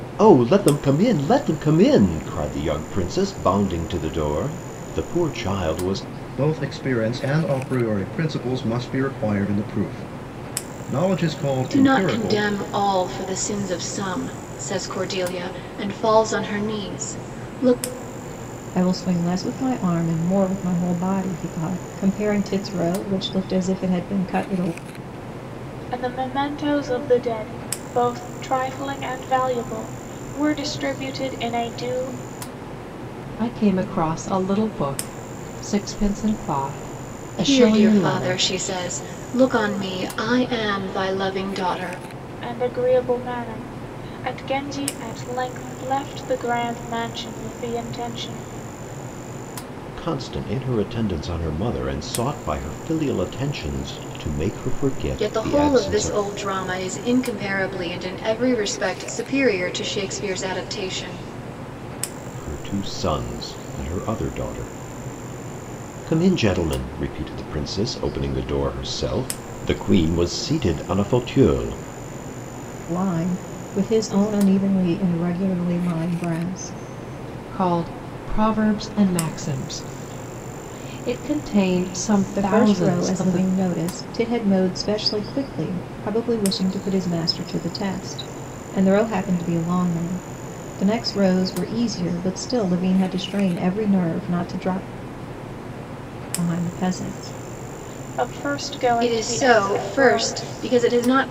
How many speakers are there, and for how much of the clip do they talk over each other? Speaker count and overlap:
six, about 5%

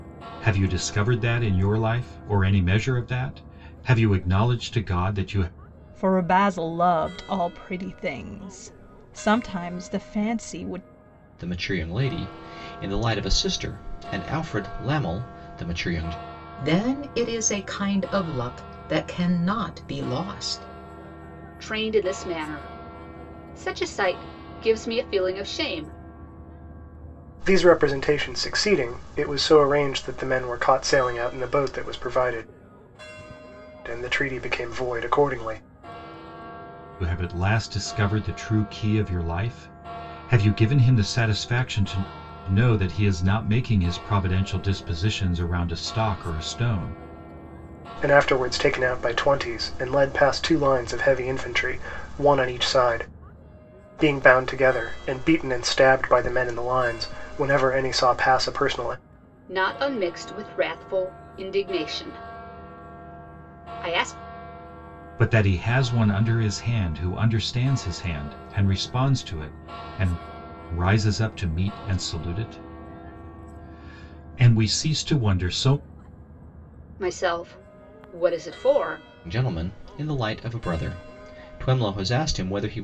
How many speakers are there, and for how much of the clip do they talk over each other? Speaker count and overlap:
six, no overlap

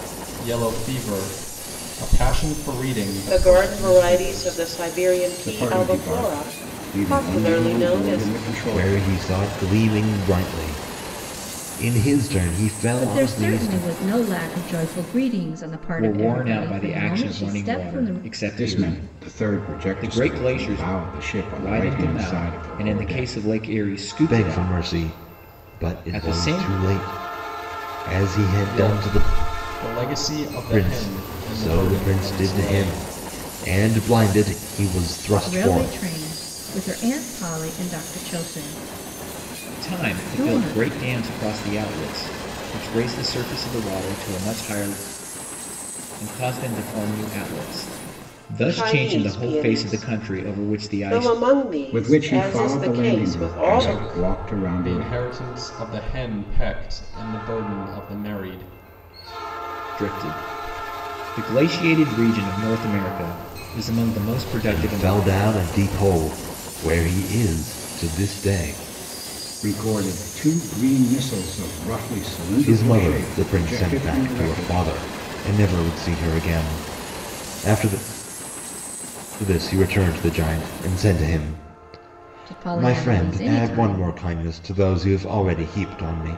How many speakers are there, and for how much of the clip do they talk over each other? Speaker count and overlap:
six, about 35%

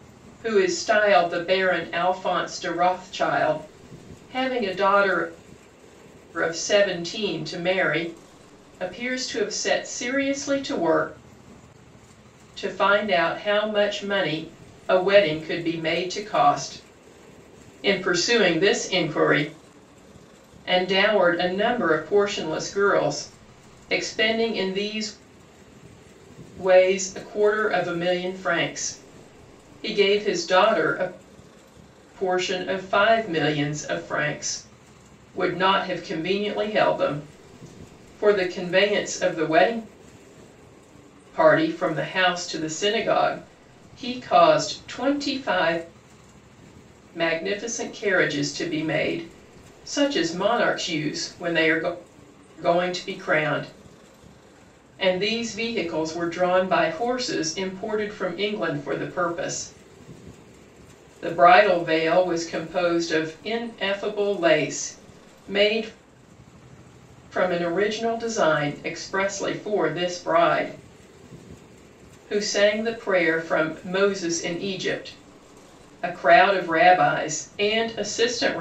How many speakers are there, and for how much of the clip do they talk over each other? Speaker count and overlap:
one, no overlap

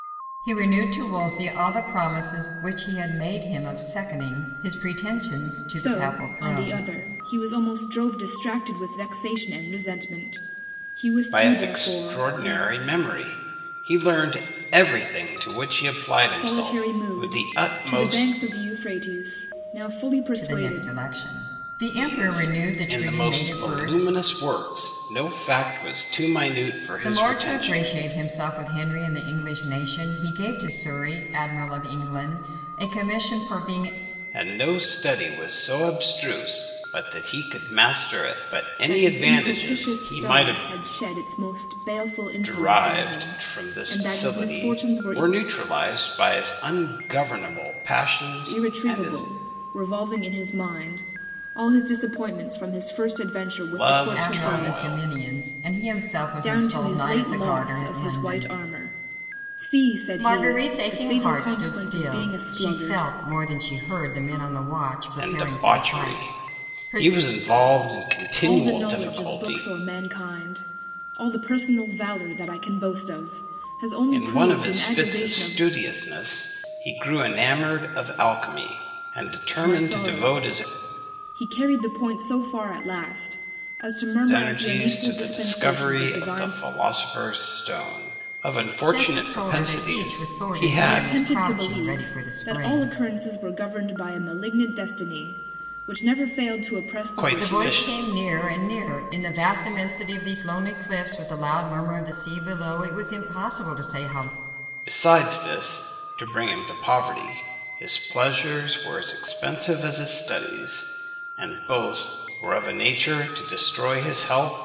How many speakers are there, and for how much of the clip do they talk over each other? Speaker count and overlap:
three, about 29%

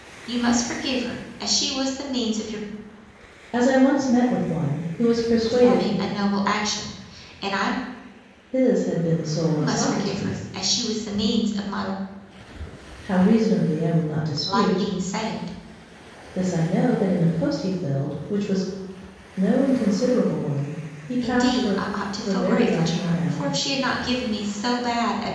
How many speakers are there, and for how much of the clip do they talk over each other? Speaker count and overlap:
two, about 15%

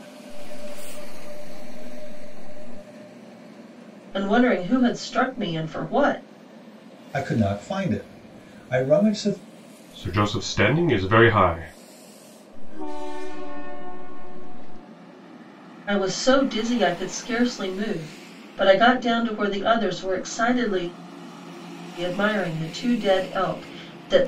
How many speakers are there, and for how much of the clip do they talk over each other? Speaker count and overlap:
four, no overlap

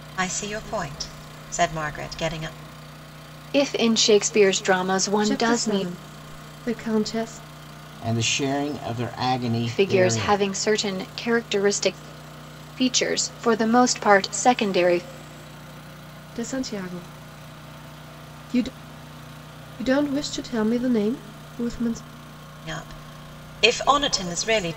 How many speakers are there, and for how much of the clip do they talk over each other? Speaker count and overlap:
four, about 6%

